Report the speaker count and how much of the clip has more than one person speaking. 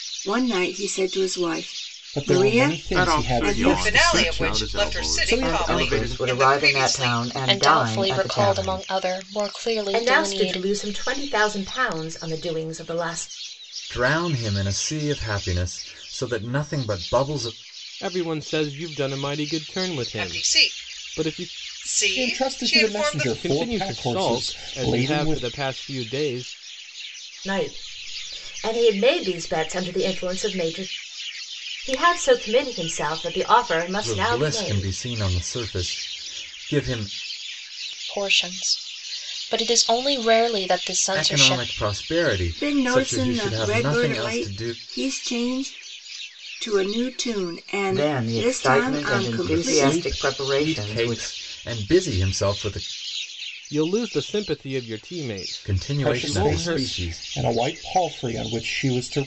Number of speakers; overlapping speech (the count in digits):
9, about 36%